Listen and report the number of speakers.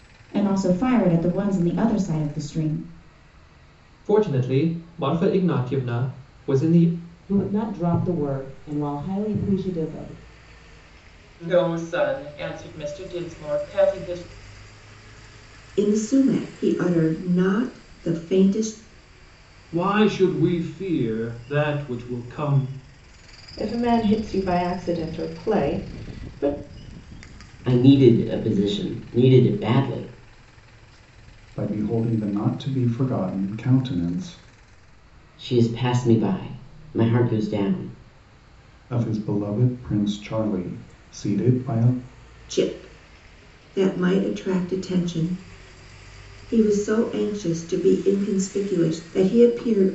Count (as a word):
nine